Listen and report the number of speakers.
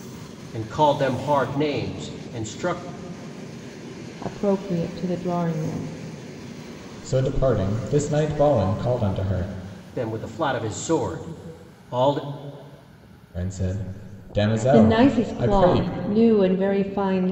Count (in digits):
3